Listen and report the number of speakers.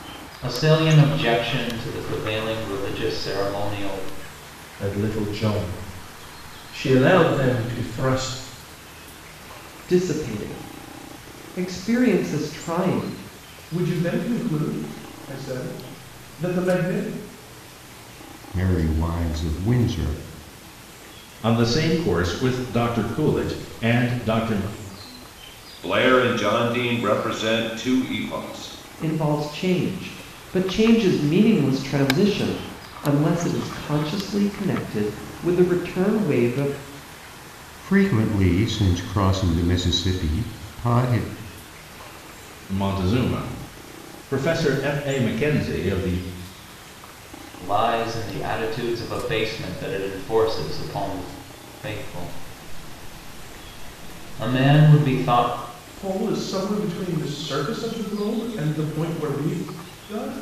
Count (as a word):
seven